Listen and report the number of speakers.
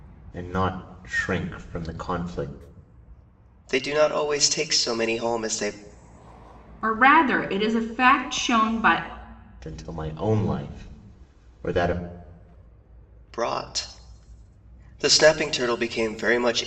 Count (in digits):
3